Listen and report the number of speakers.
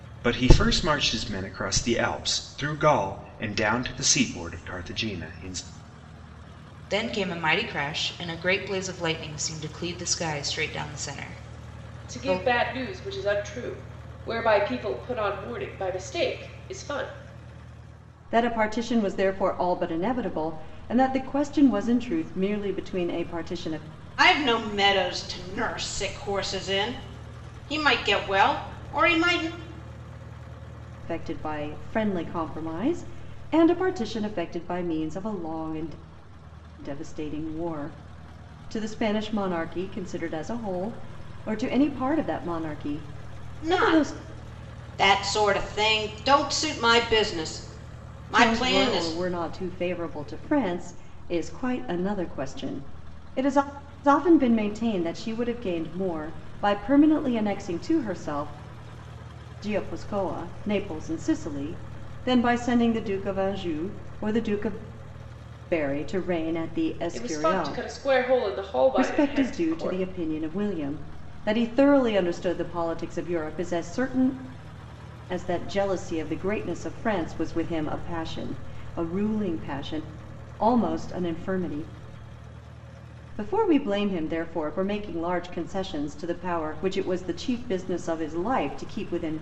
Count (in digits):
5